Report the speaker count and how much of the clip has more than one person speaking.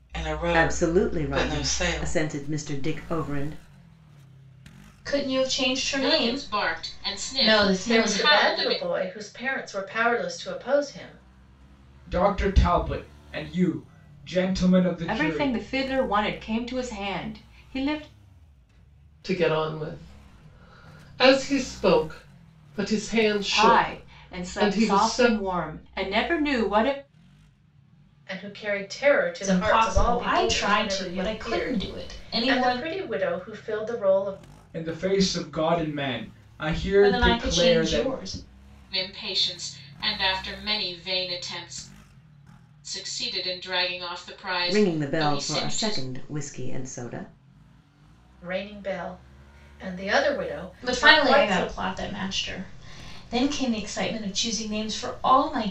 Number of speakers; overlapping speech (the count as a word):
eight, about 24%